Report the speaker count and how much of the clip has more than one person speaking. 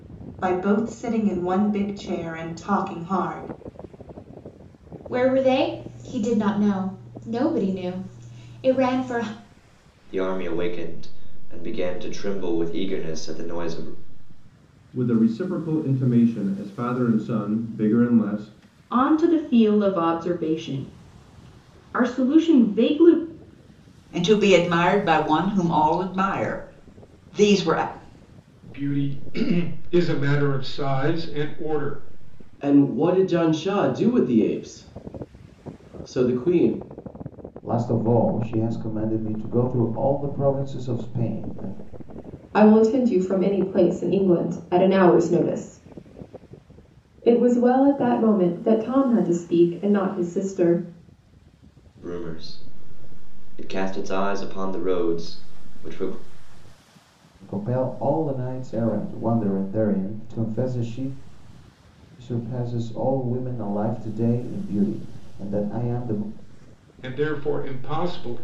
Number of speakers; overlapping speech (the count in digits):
10, no overlap